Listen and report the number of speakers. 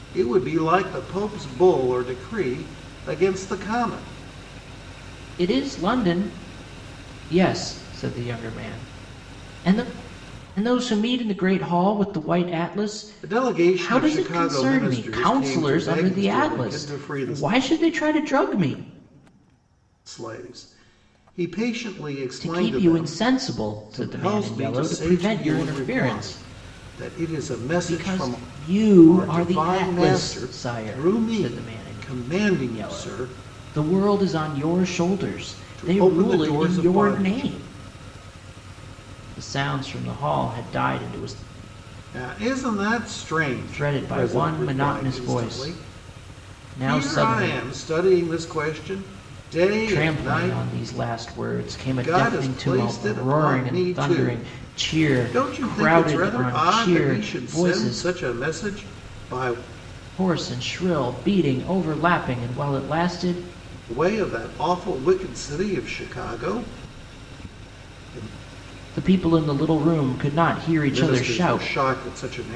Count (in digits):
2